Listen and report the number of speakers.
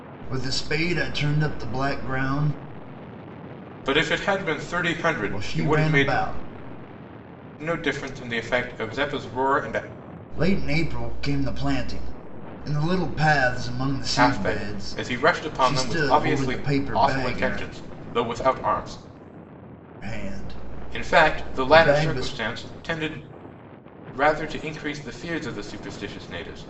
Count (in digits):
2